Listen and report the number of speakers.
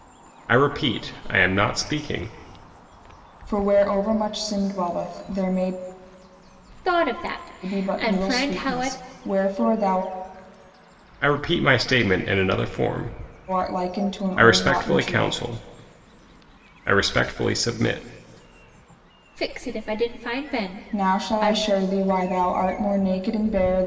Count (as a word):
three